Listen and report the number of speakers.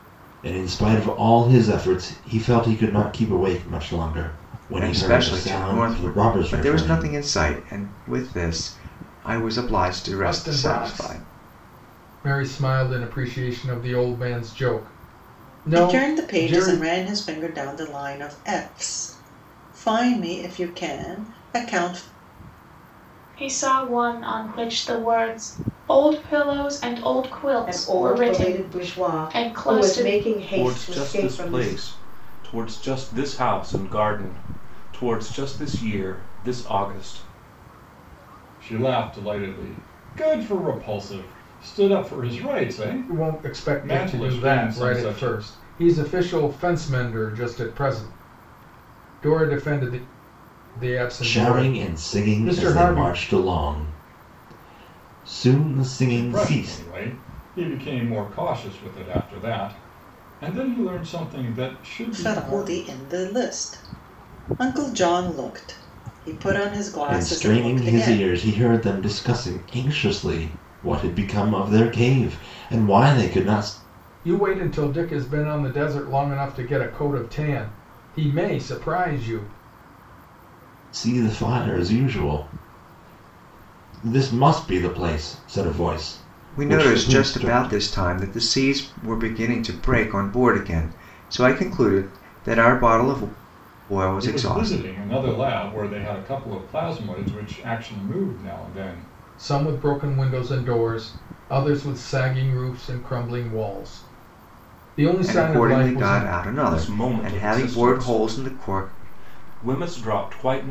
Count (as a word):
eight